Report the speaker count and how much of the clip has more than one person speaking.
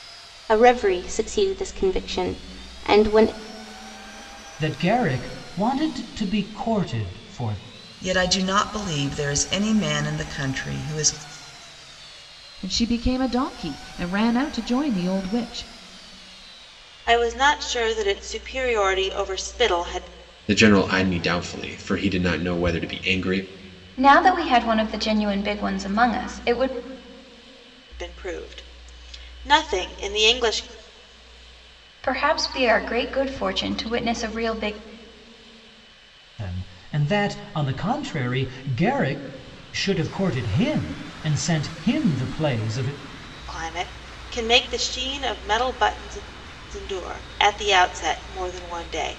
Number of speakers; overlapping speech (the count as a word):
seven, no overlap